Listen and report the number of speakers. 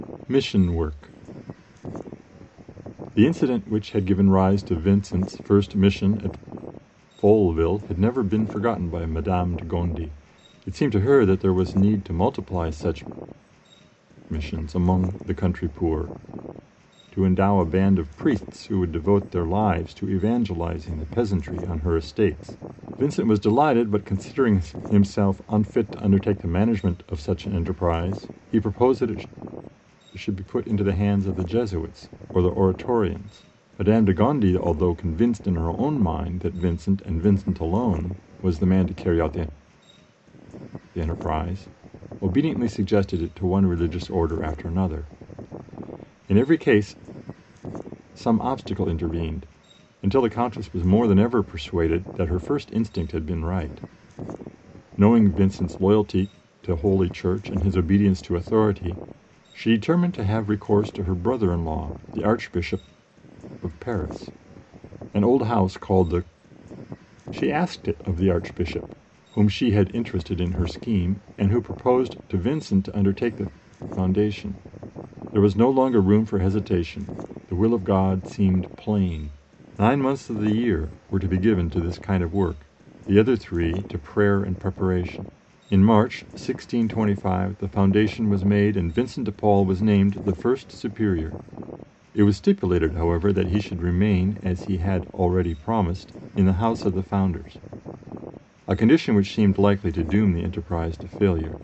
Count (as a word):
one